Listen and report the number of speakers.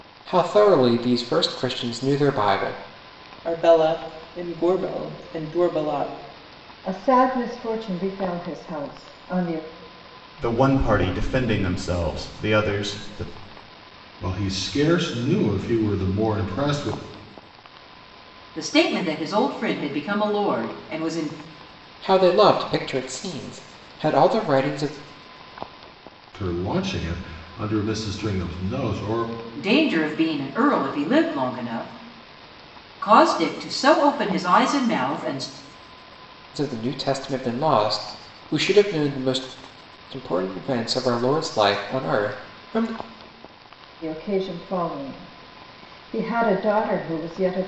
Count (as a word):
six